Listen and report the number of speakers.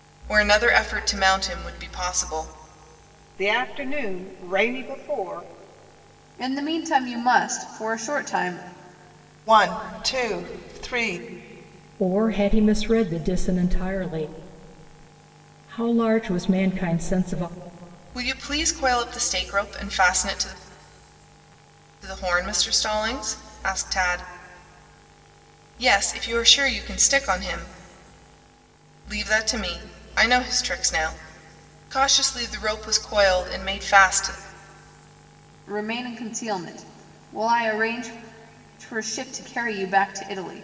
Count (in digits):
5